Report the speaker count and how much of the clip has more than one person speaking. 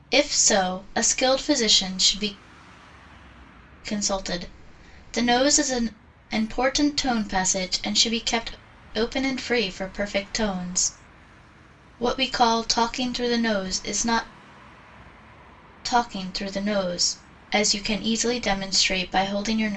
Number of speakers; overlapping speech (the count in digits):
1, no overlap